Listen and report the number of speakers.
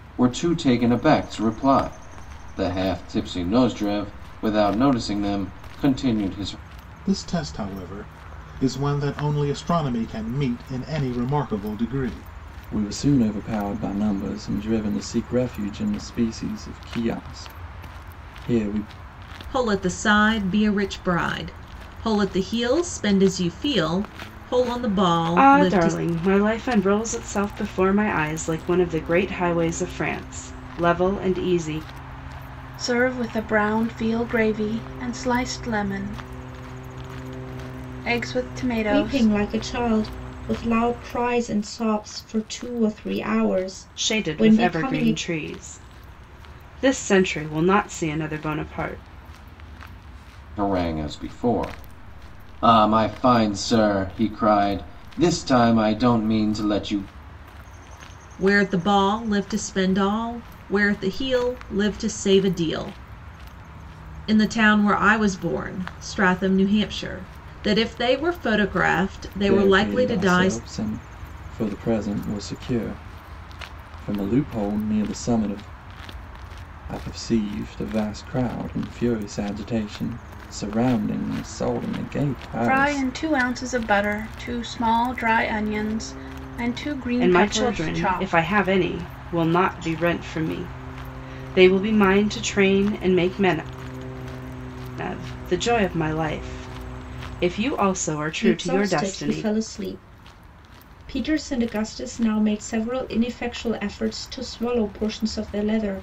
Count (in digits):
7